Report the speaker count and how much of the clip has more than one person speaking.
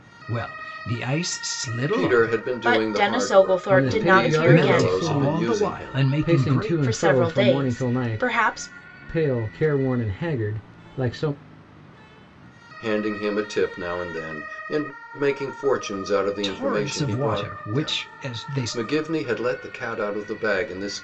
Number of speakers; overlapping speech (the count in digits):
4, about 40%